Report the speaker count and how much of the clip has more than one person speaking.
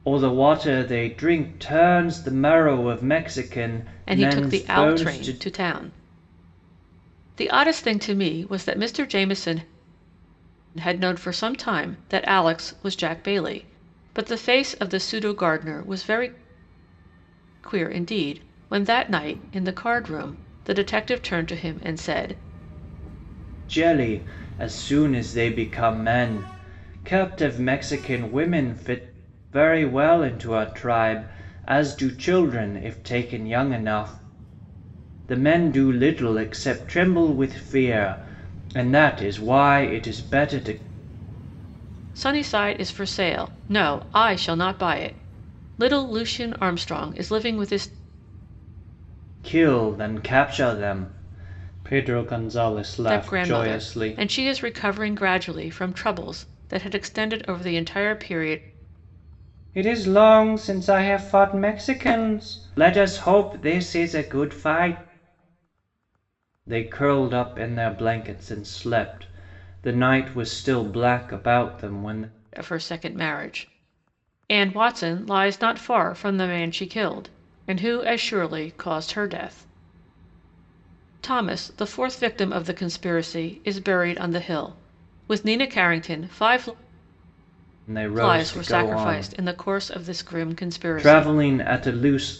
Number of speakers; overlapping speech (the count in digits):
2, about 4%